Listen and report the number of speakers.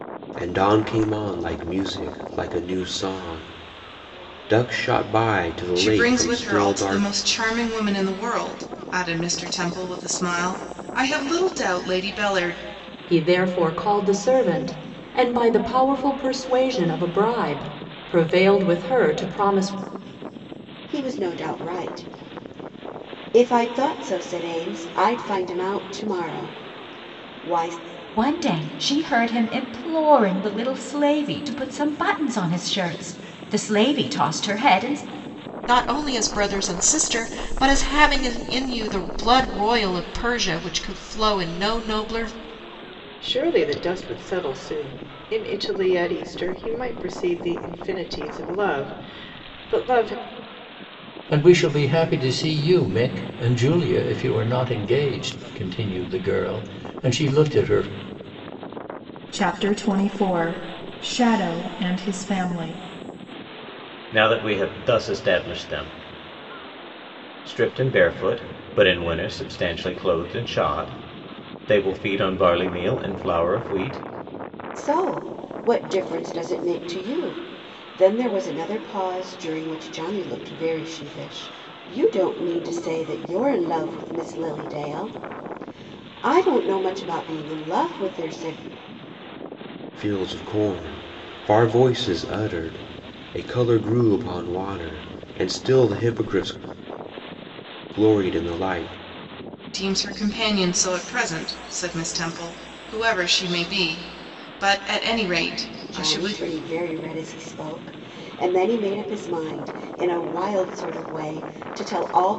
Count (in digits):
10